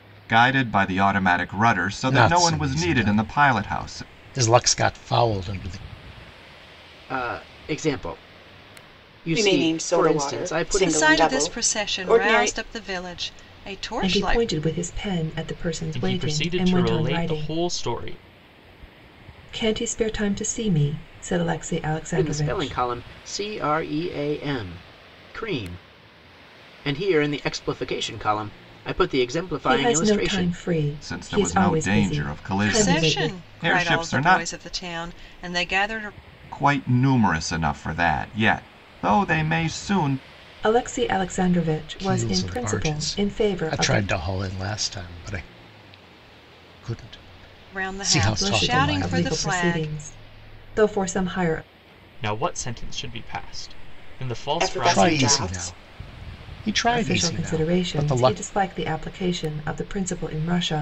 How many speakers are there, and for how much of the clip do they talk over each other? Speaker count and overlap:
7, about 32%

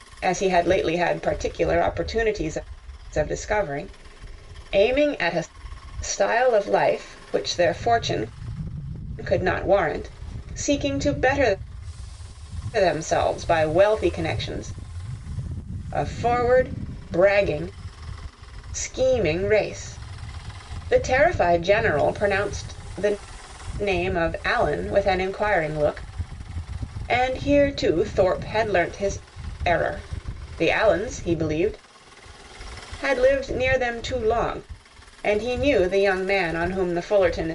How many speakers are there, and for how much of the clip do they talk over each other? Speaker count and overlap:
1, no overlap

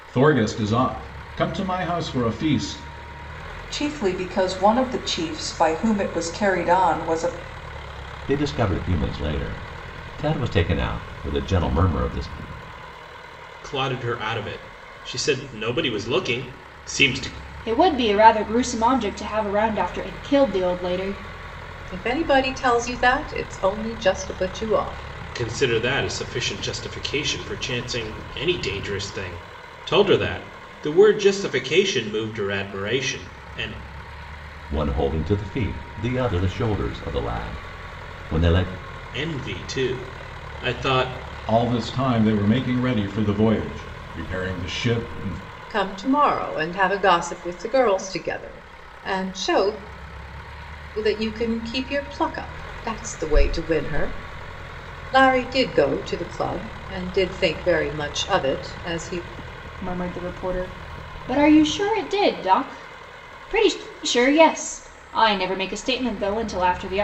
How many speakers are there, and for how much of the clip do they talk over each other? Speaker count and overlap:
6, no overlap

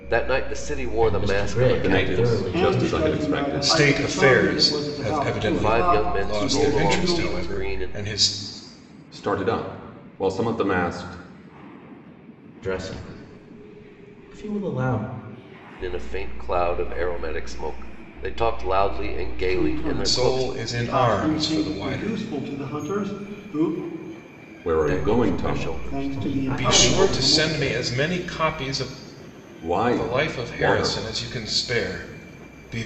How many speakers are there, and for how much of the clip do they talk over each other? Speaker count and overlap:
5, about 42%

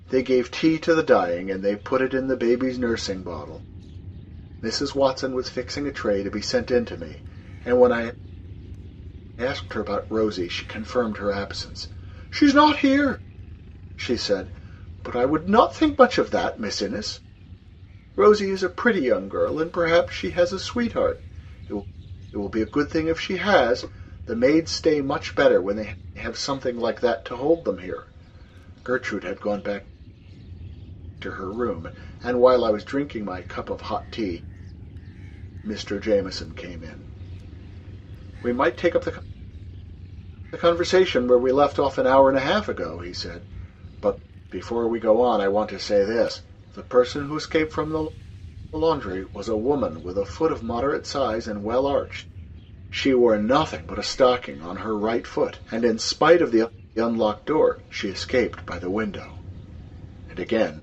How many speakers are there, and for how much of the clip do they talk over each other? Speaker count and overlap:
1, no overlap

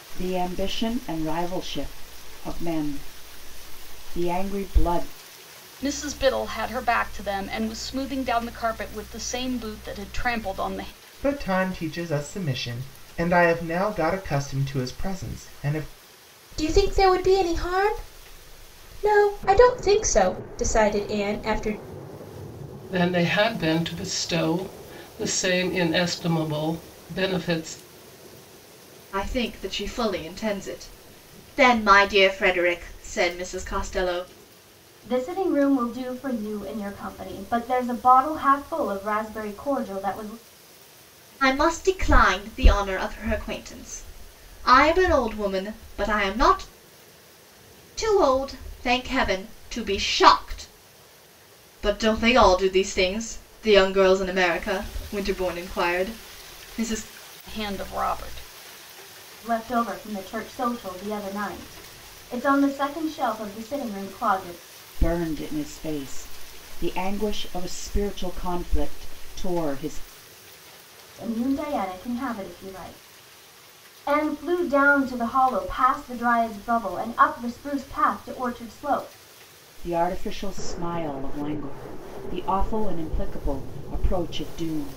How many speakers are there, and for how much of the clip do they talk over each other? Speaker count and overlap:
7, no overlap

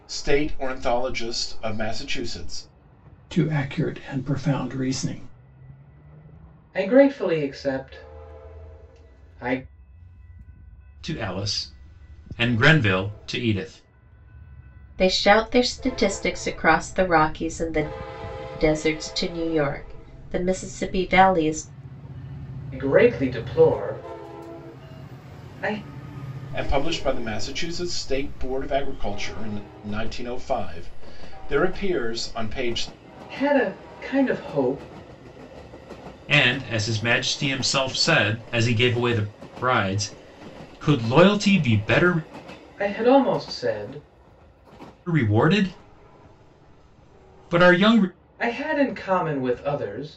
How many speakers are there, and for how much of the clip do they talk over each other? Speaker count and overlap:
5, no overlap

